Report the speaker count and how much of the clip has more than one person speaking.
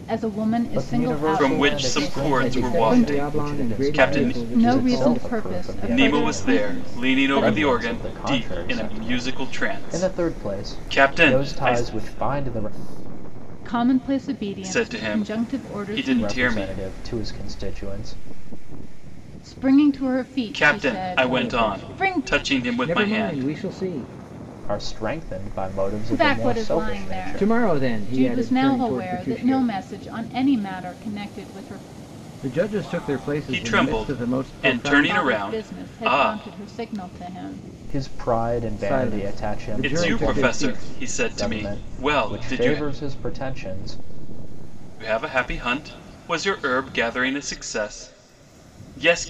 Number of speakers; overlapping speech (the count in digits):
4, about 53%